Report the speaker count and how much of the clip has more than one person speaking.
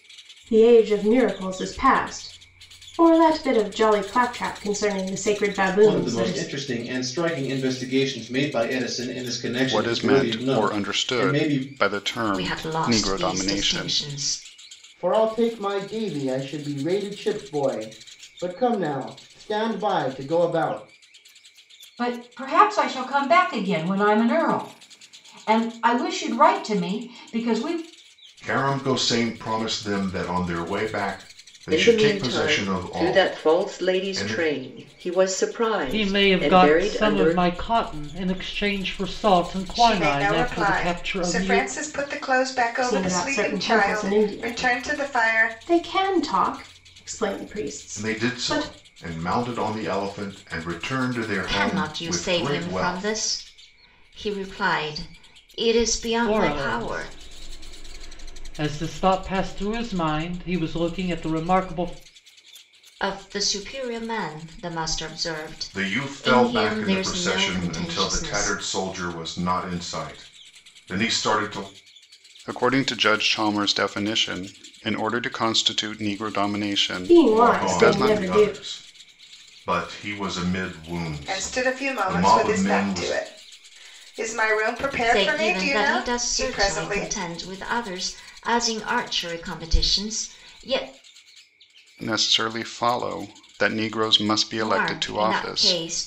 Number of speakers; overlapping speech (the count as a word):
ten, about 27%